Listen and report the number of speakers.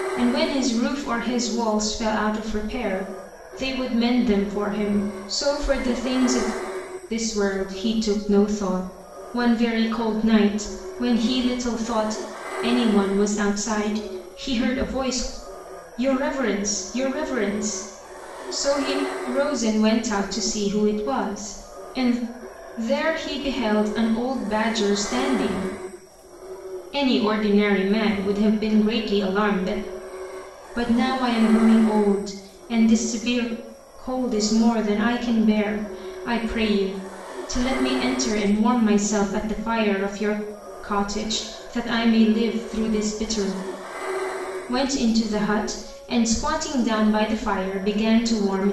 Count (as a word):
one